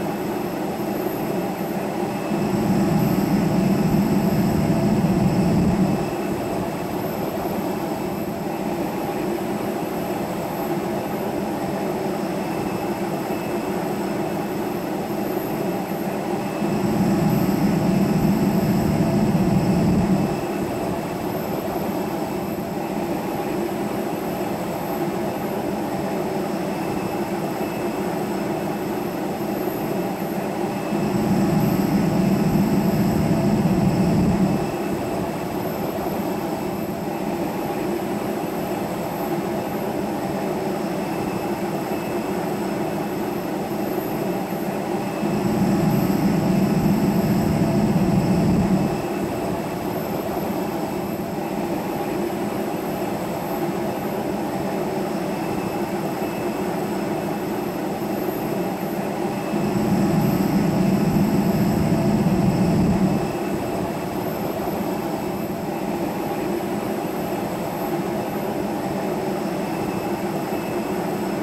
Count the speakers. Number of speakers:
zero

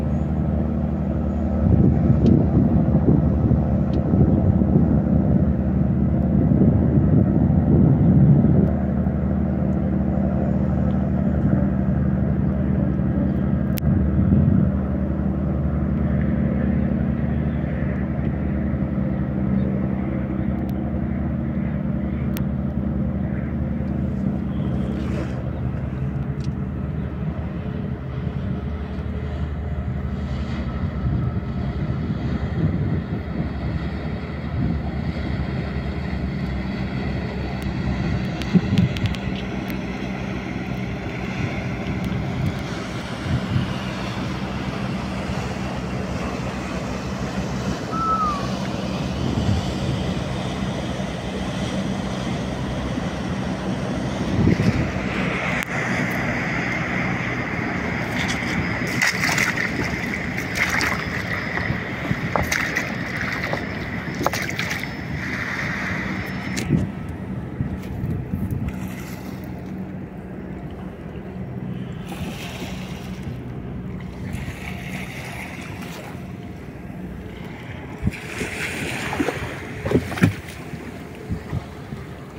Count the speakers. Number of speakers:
zero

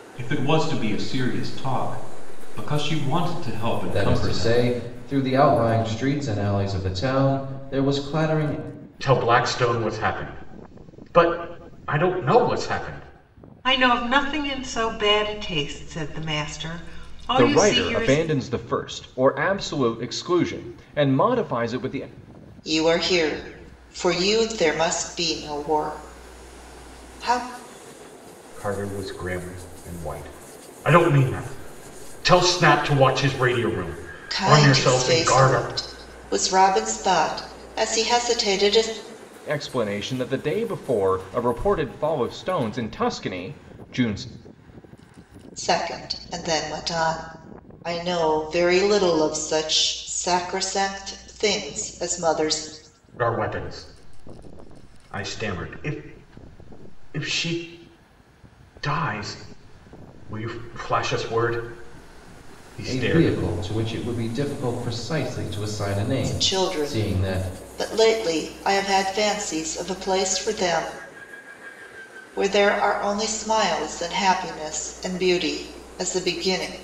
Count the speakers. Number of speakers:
six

